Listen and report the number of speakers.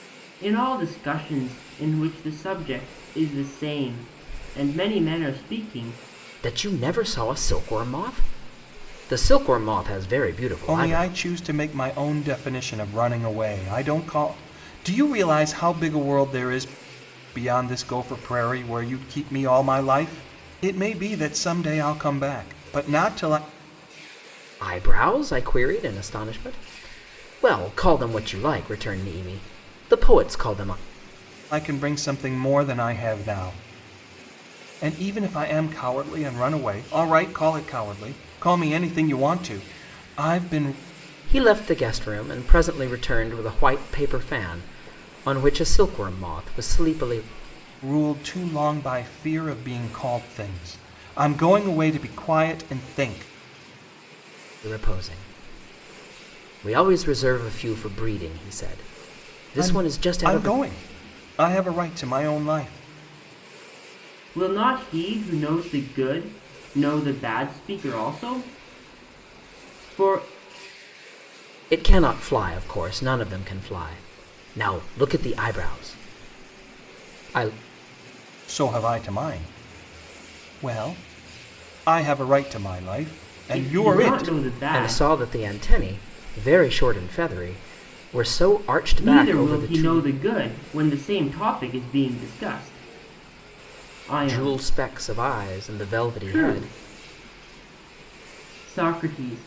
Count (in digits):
3